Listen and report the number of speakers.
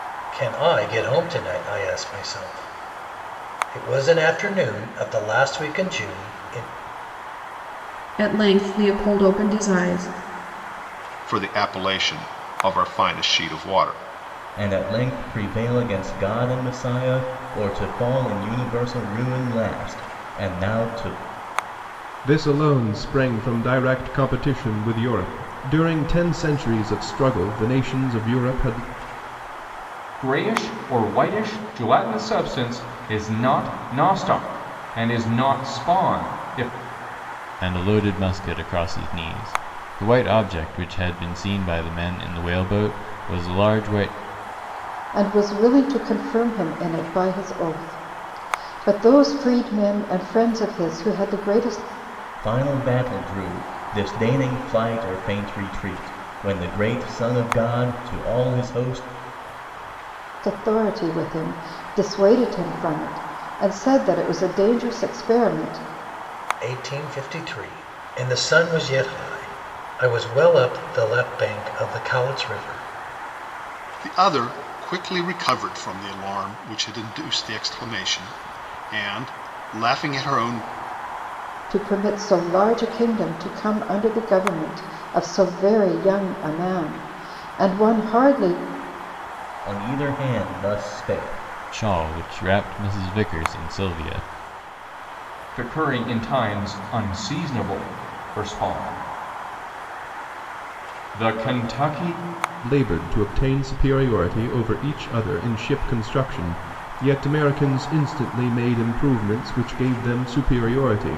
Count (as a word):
eight